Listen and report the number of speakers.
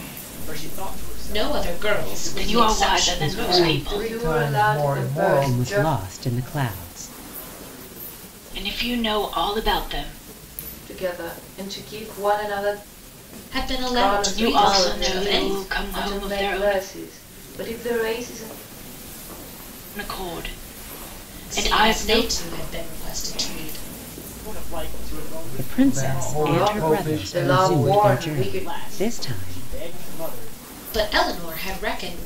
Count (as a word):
six